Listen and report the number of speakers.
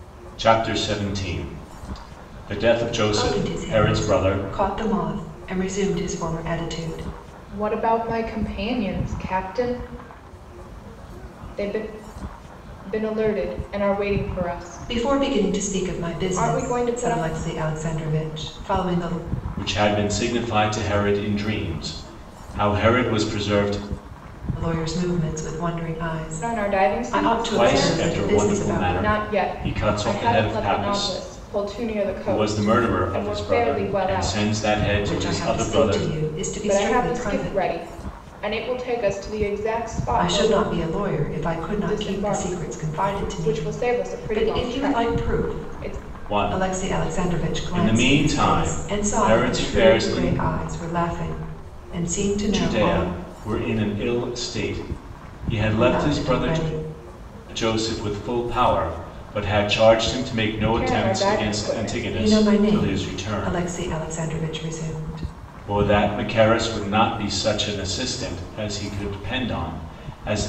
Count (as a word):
three